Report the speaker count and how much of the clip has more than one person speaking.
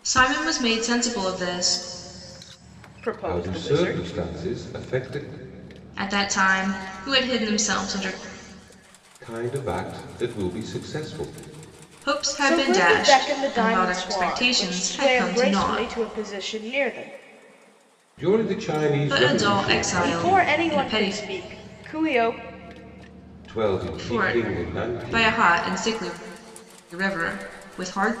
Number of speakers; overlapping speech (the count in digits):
3, about 29%